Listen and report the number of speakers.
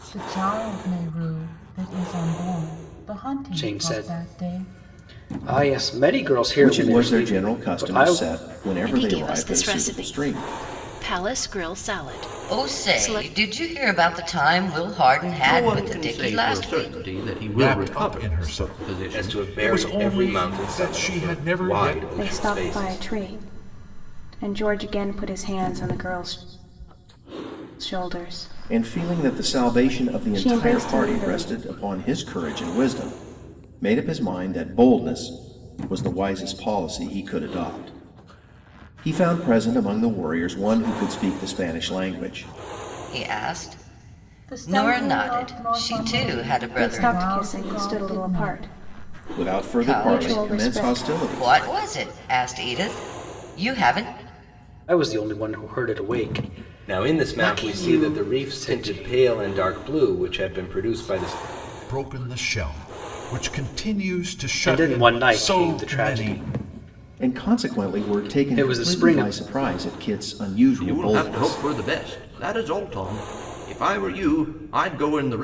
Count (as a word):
nine